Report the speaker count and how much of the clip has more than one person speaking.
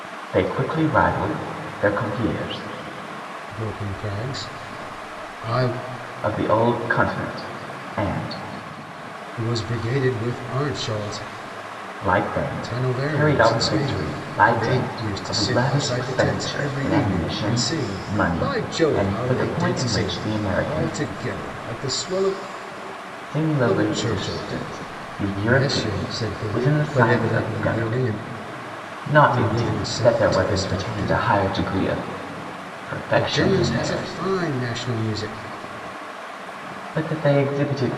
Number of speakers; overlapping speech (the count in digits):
2, about 42%